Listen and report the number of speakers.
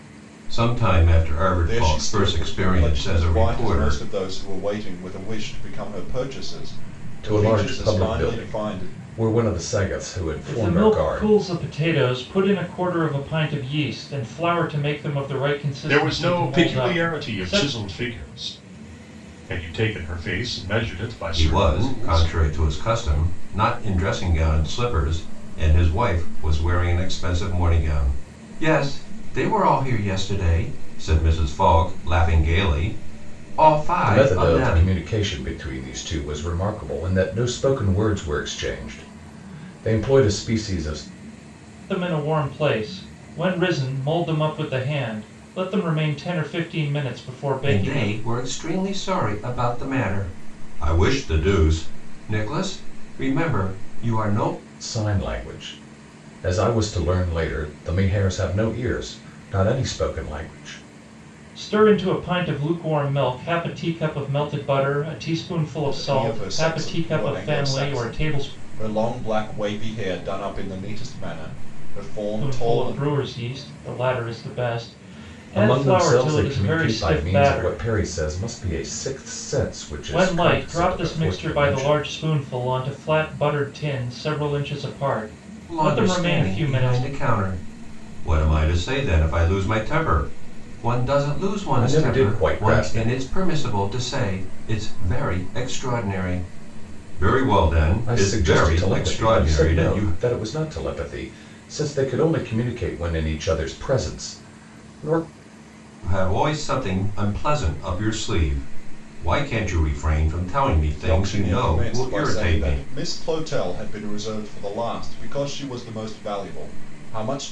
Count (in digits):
5